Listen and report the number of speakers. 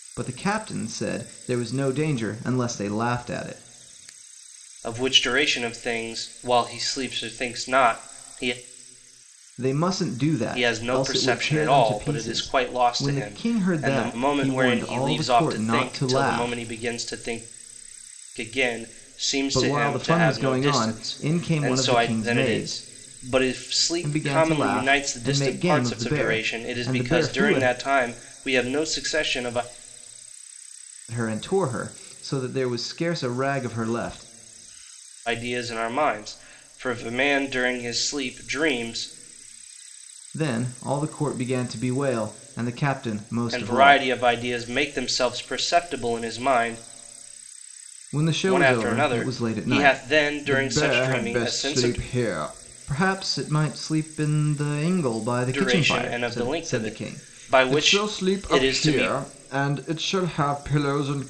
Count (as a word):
two